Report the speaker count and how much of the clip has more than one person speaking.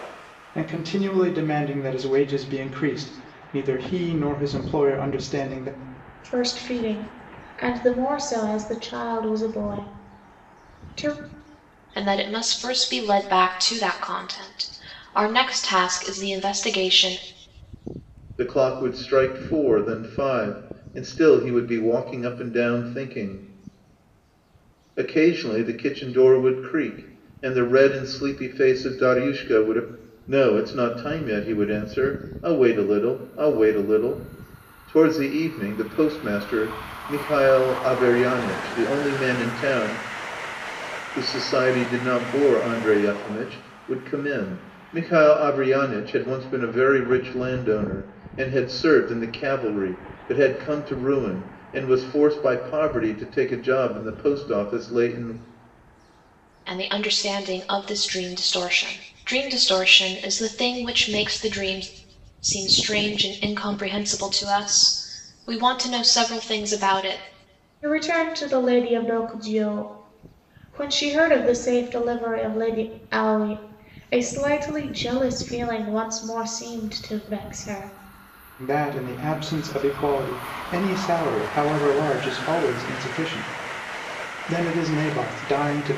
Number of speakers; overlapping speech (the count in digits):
4, no overlap